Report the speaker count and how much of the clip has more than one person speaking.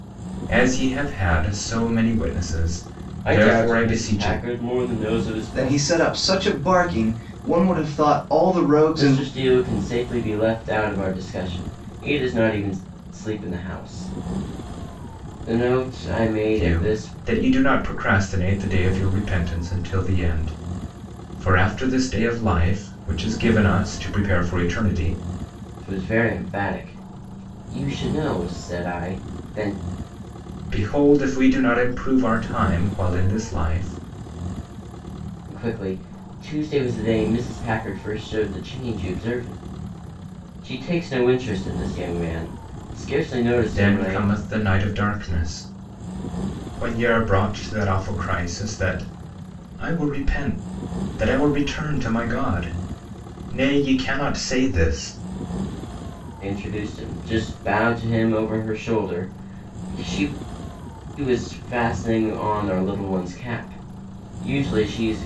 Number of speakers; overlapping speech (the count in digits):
3, about 5%